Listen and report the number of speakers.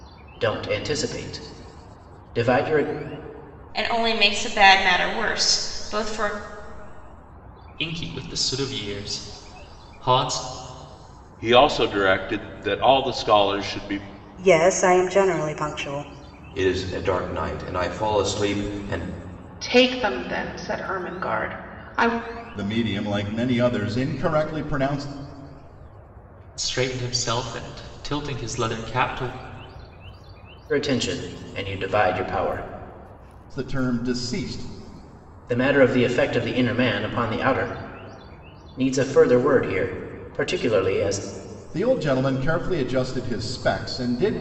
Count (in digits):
8